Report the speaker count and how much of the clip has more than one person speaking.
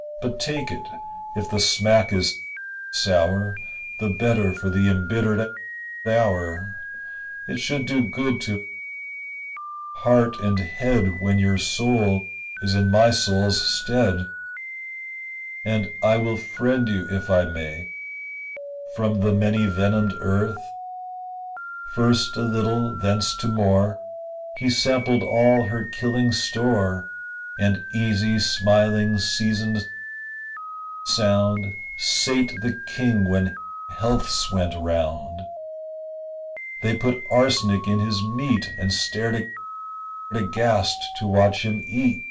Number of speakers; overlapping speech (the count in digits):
1, no overlap